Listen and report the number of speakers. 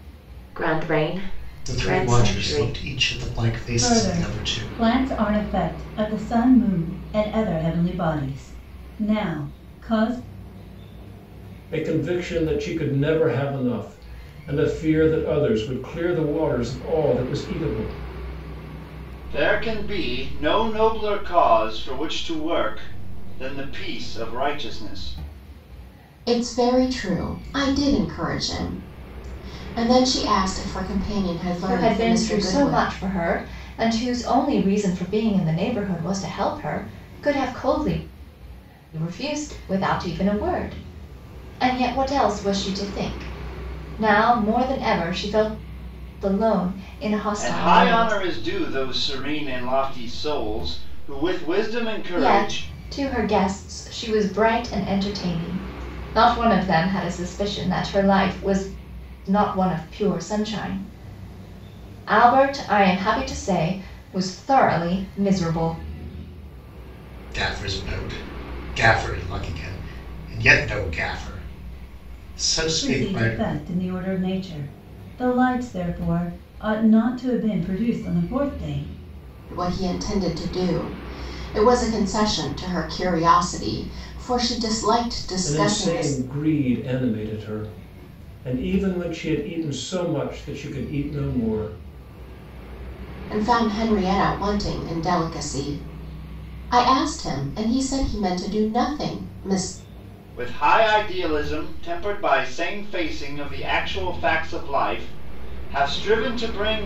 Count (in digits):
7